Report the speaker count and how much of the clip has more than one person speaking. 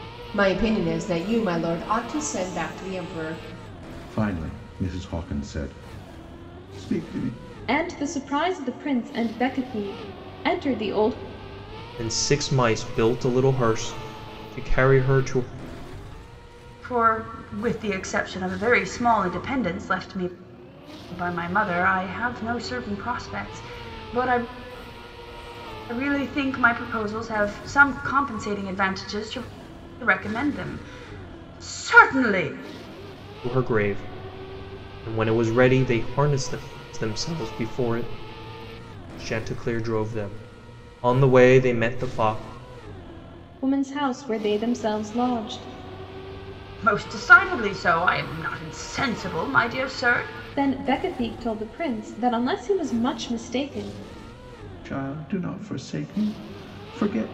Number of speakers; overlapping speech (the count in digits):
5, no overlap